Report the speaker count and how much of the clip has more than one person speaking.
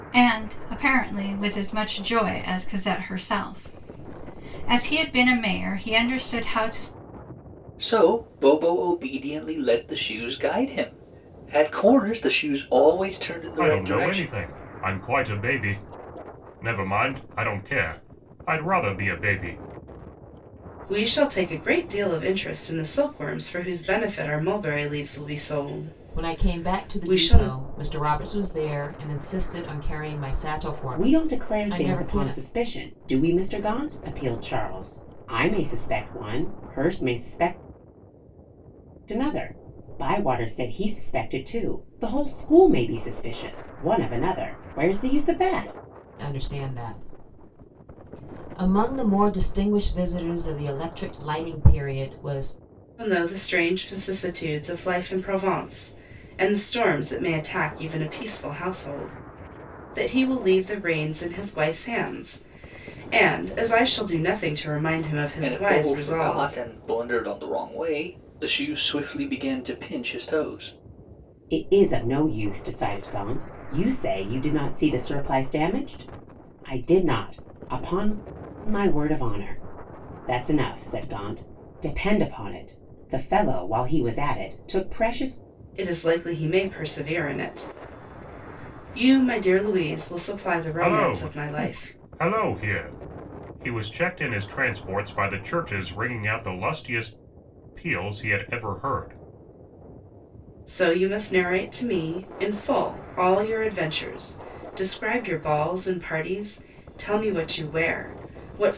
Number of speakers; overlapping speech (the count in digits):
6, about 6%